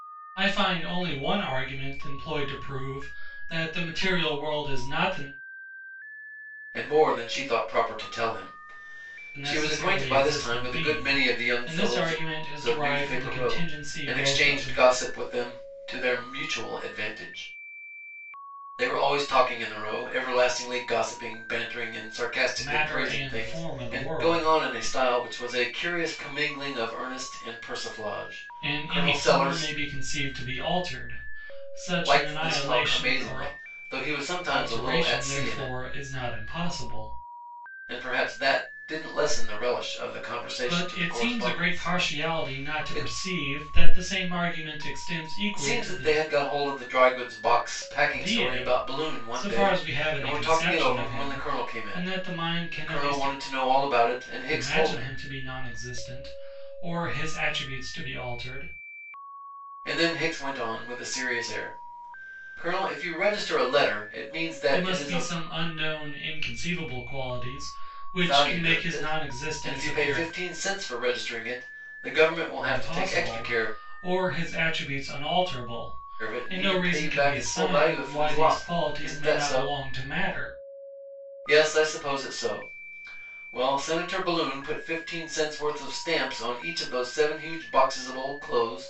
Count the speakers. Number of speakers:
2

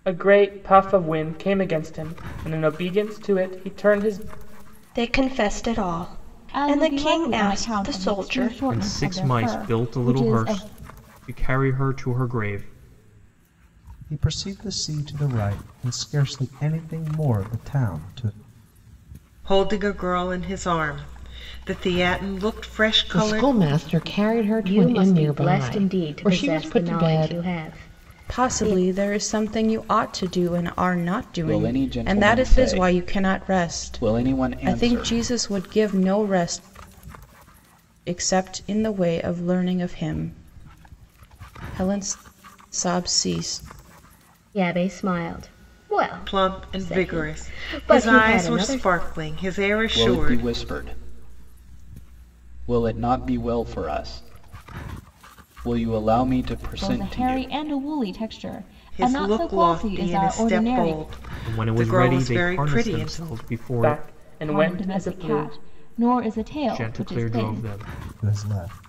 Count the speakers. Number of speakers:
10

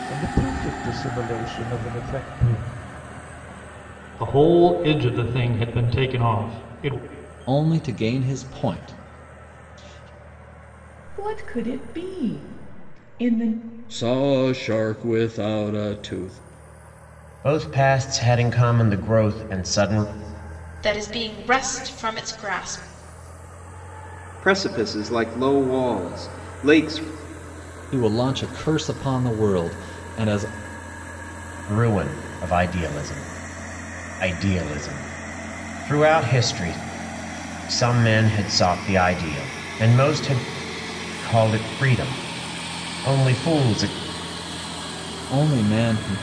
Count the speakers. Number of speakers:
8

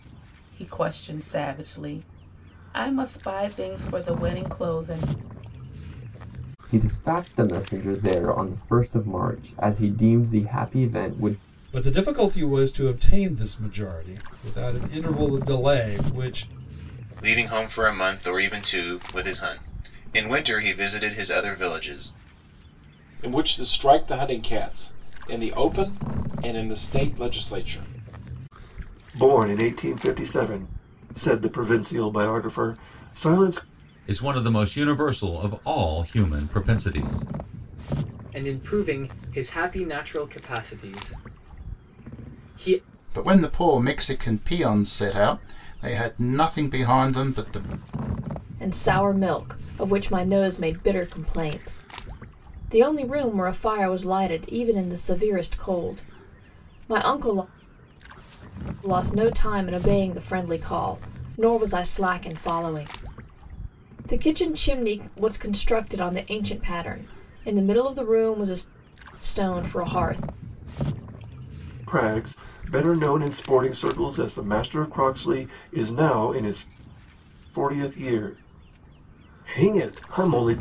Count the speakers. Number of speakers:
10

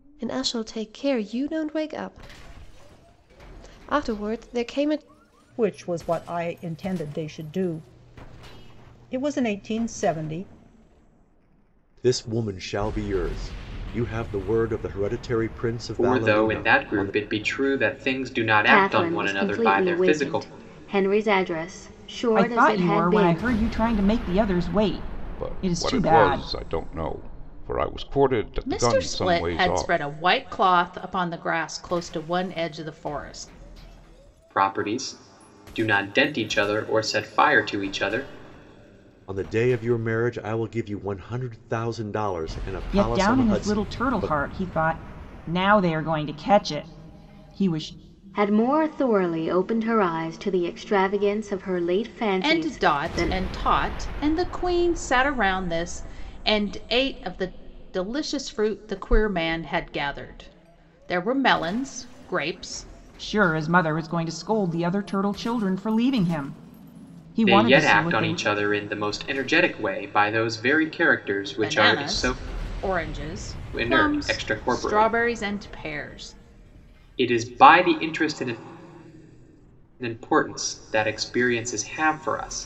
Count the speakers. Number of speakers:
8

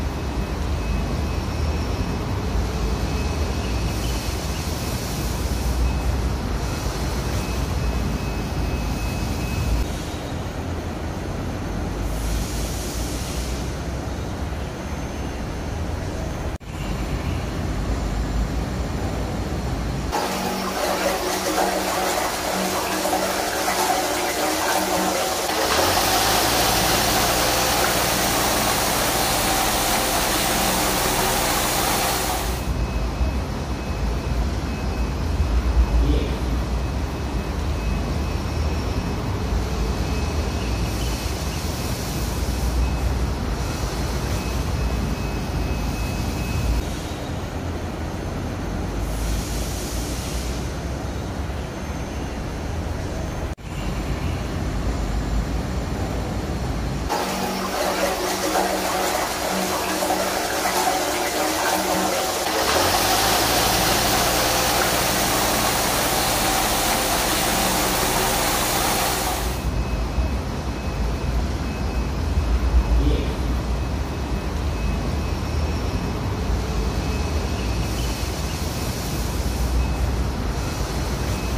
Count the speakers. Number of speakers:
0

